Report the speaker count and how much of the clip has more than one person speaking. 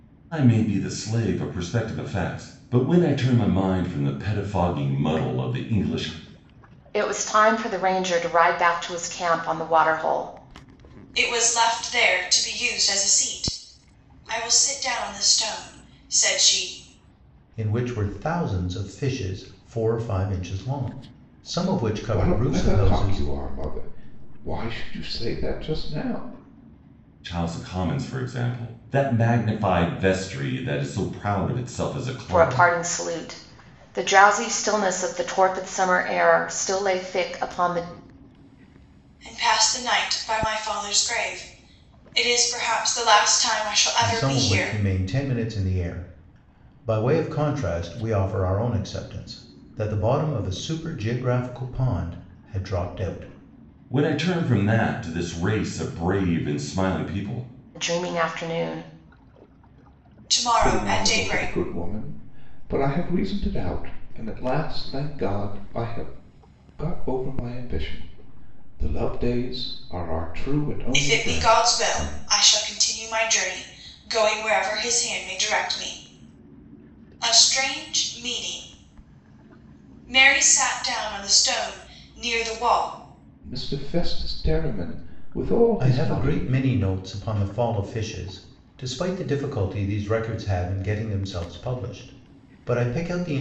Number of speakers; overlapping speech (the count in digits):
5, about 6%